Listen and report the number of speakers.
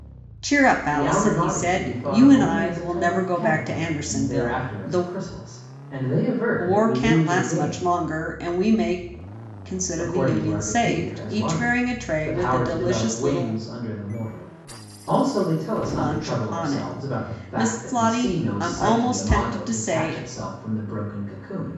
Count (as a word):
two